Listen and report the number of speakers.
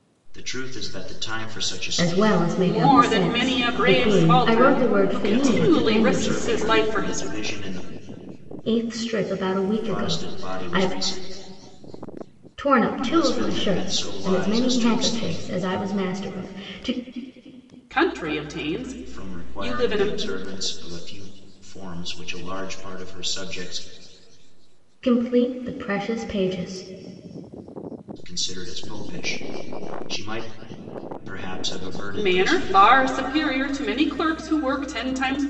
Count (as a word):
three